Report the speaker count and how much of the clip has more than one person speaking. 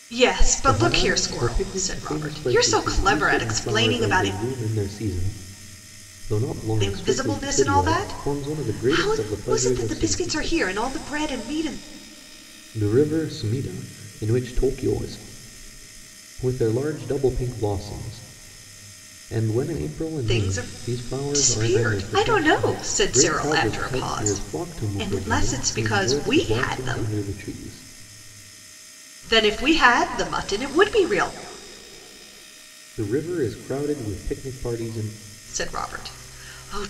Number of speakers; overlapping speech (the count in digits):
2, about 37%